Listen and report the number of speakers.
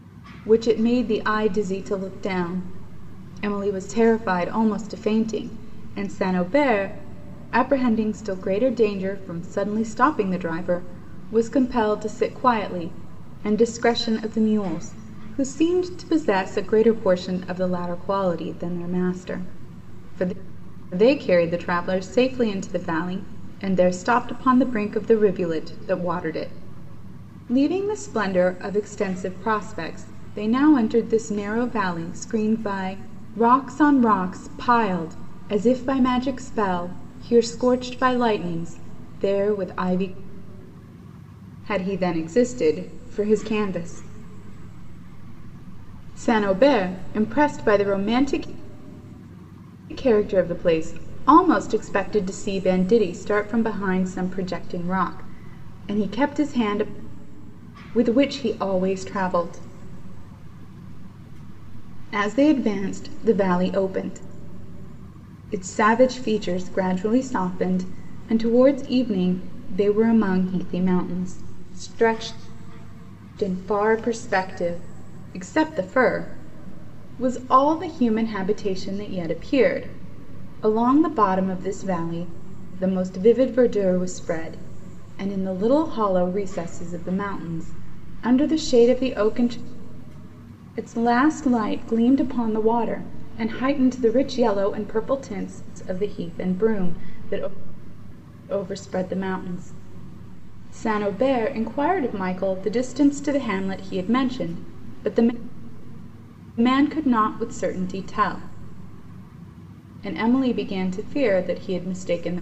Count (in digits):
1